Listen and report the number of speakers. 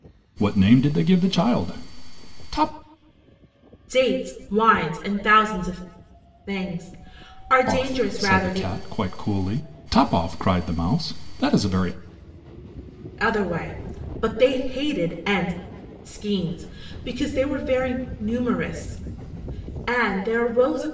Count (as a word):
two